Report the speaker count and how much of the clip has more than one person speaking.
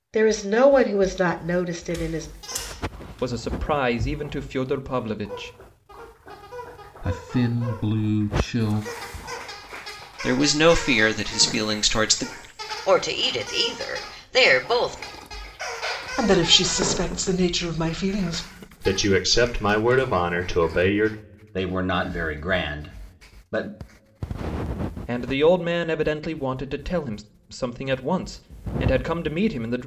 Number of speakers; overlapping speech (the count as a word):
eight, no overlap